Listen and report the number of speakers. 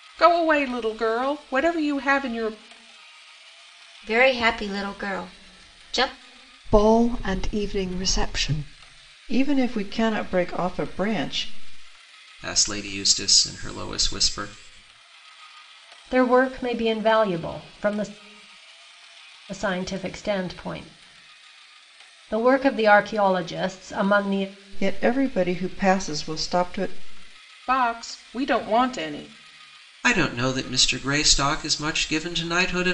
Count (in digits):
6